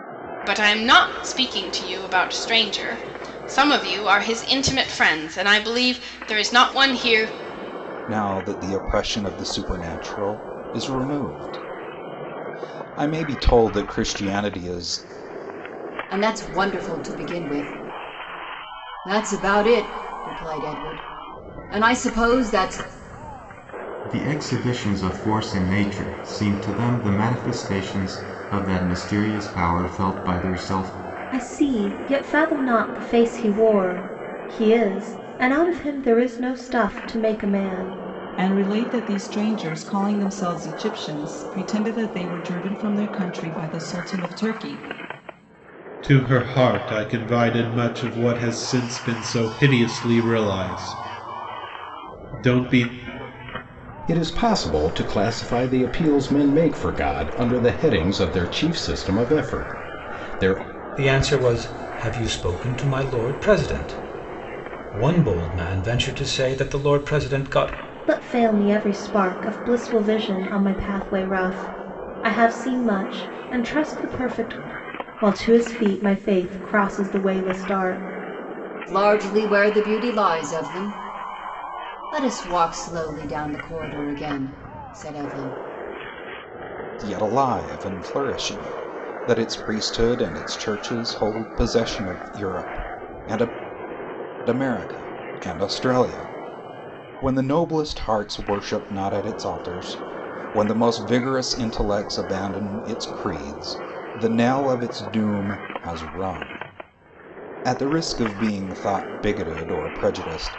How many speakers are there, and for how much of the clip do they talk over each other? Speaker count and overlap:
nine, no overlap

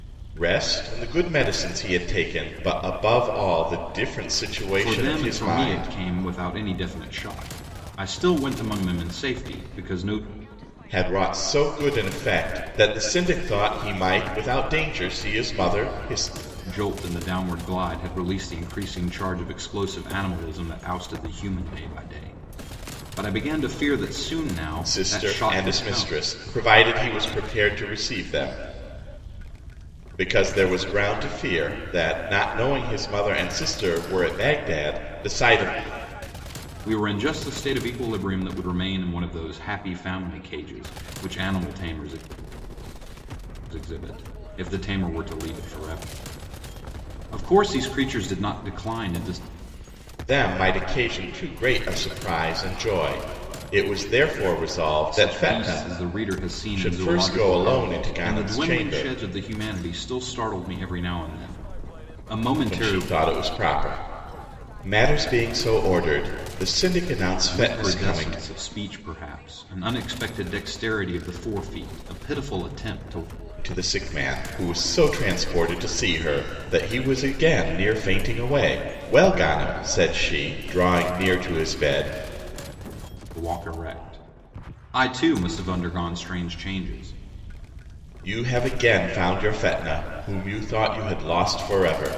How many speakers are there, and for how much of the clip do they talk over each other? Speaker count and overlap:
two, about 8%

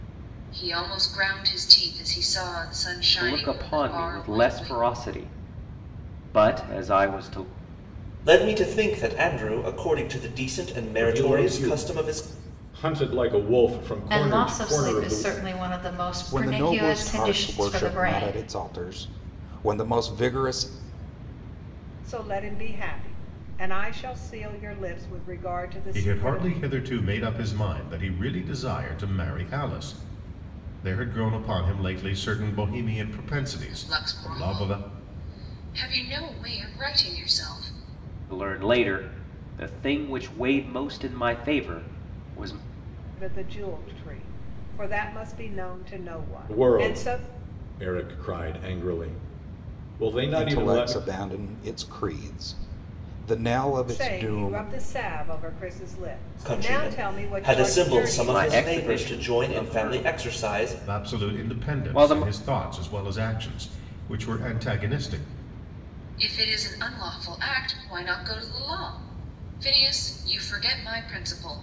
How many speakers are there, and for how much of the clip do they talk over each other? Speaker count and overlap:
eight, about 23%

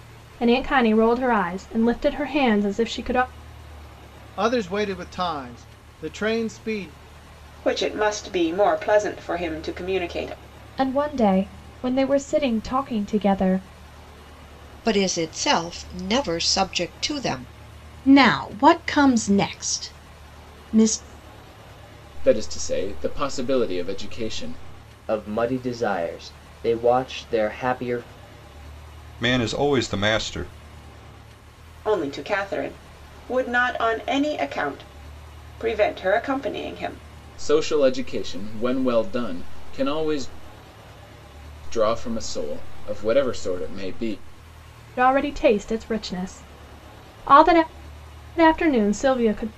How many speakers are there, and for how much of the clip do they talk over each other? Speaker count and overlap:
nine, no overlap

